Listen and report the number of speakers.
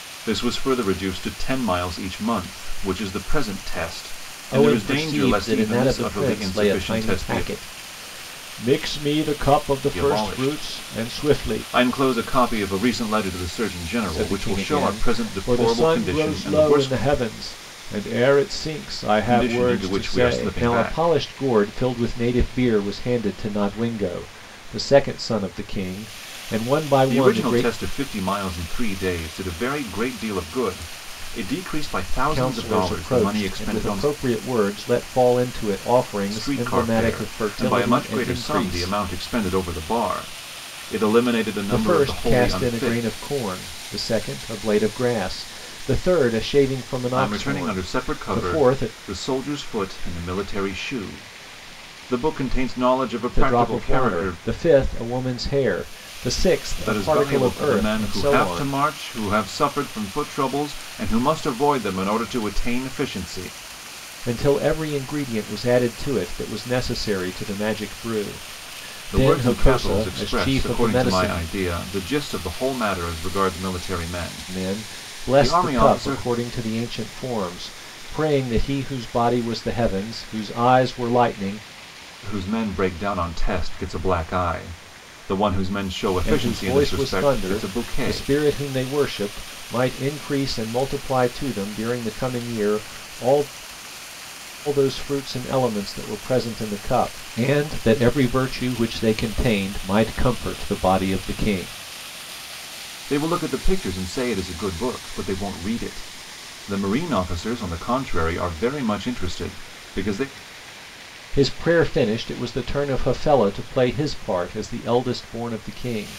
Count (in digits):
2